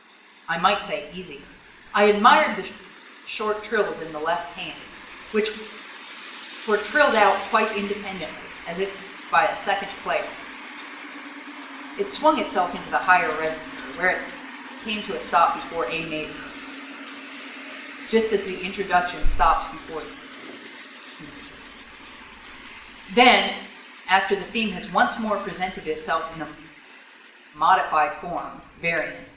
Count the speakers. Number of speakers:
1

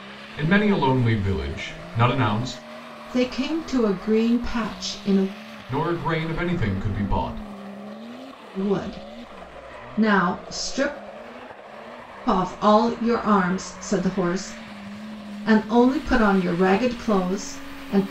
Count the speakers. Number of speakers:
2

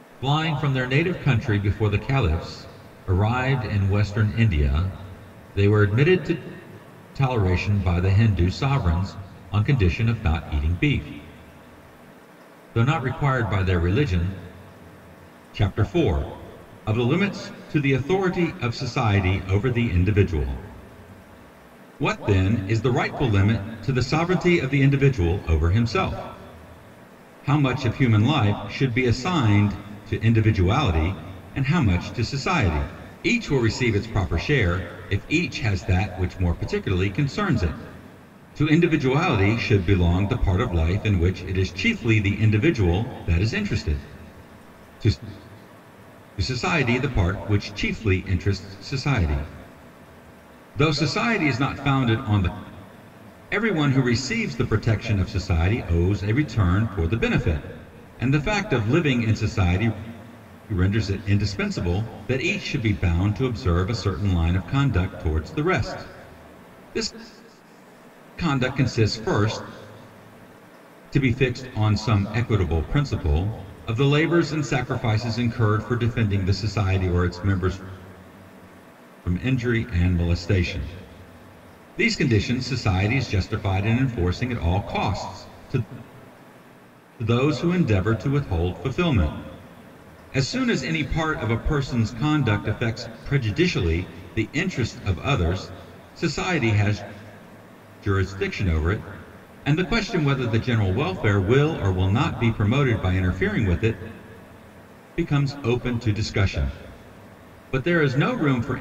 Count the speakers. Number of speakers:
1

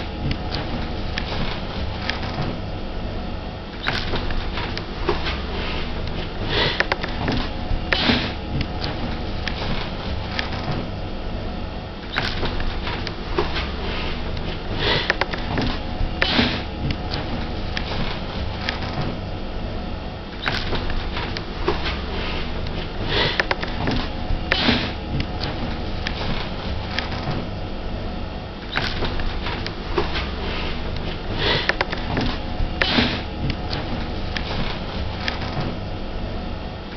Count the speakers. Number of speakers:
0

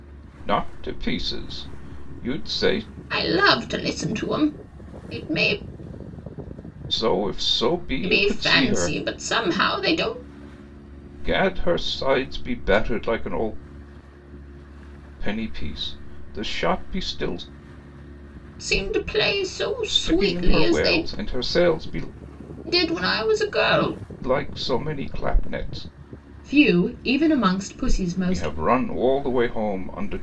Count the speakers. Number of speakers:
2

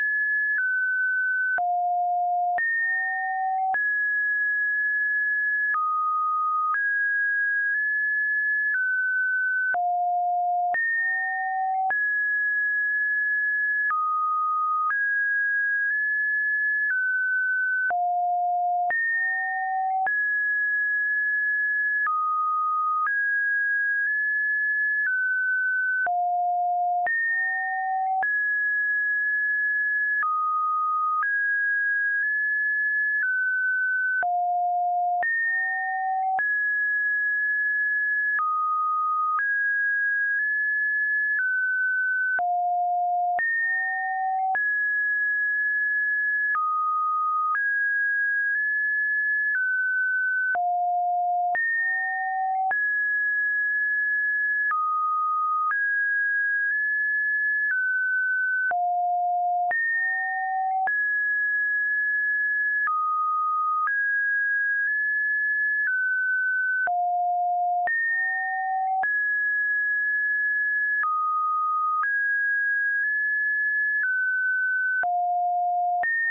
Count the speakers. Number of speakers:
0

